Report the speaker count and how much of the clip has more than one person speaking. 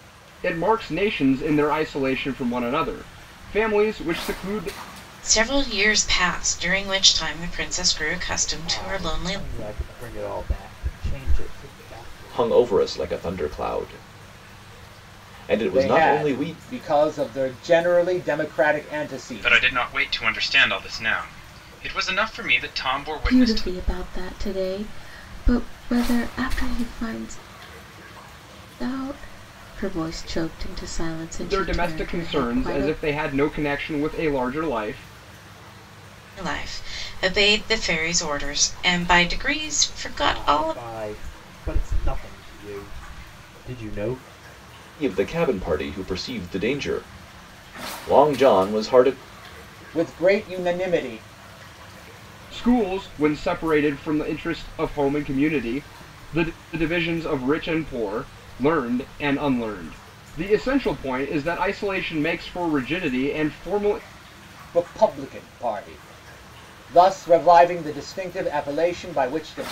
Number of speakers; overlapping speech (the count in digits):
7, about 8%